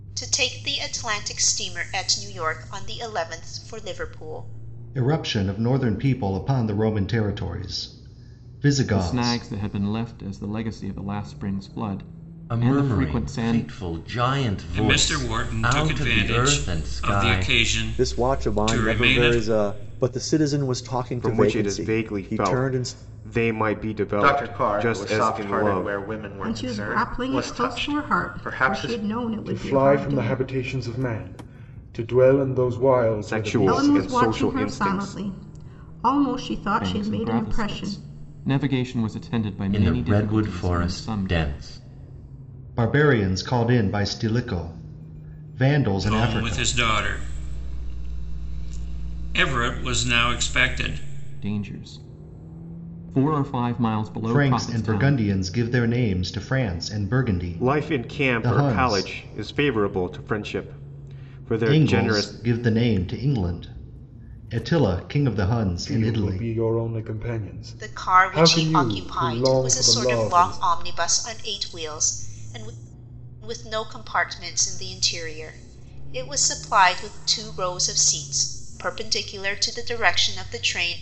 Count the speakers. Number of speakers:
10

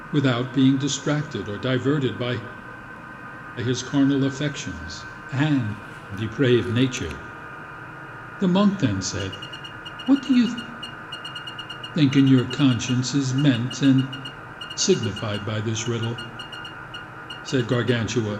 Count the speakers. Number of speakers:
1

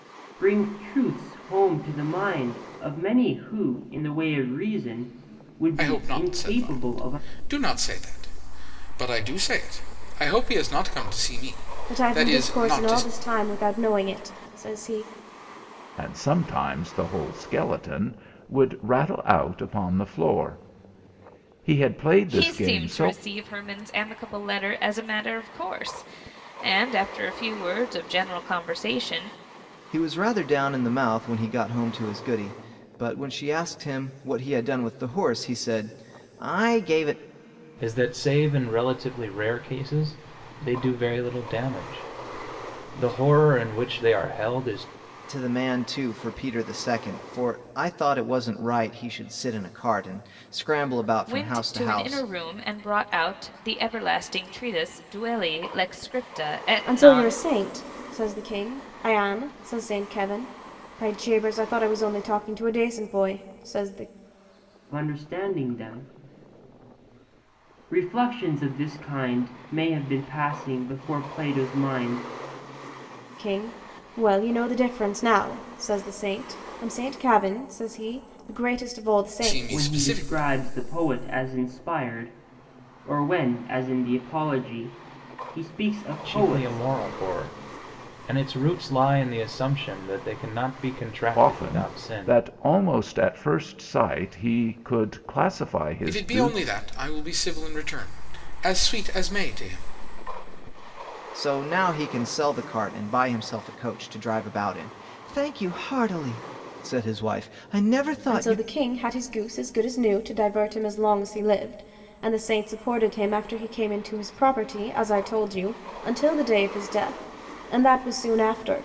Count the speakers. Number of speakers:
7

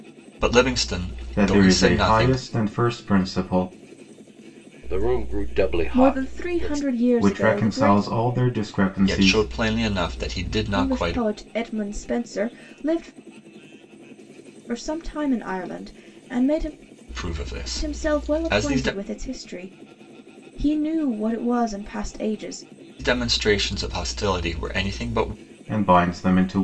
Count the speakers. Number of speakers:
4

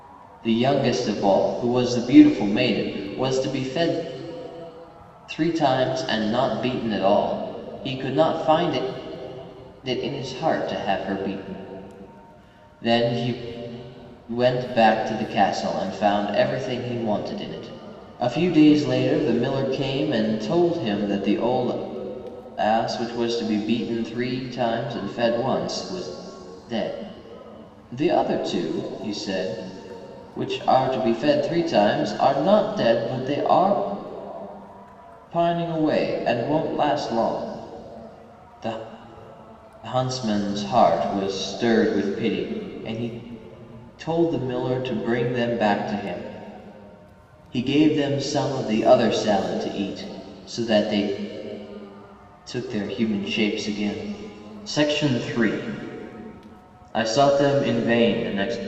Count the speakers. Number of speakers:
1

